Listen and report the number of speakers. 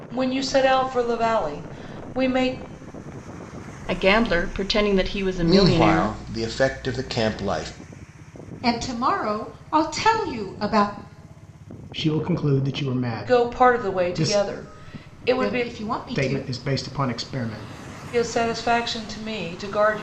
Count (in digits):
5